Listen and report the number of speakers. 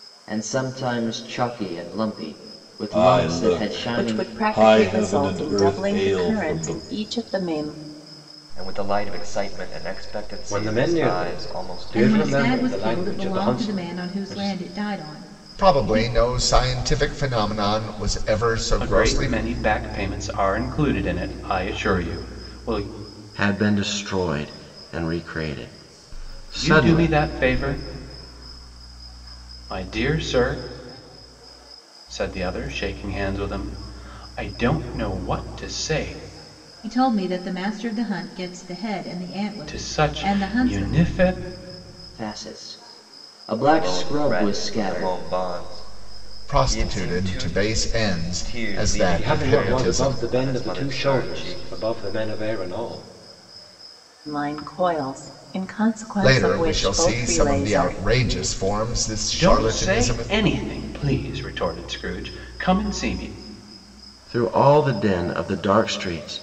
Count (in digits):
9